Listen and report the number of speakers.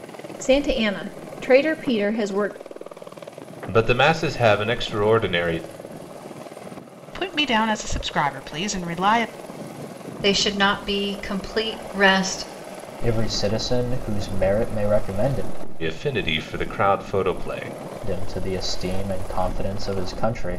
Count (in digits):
5